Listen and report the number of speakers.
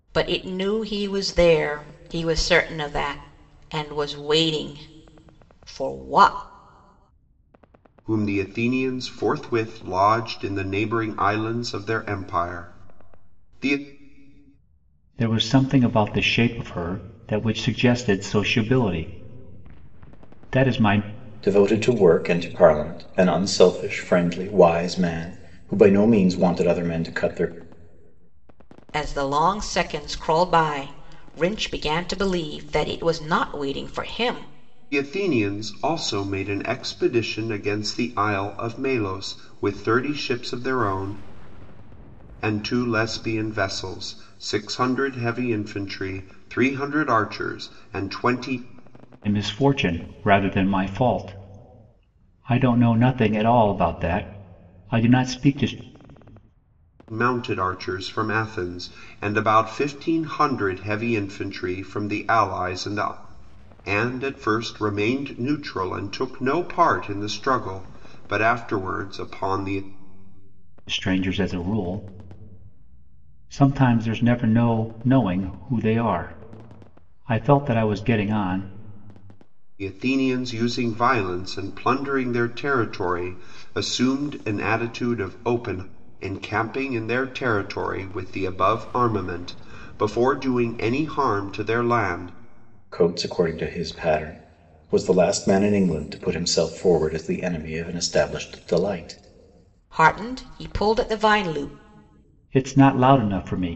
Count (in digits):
4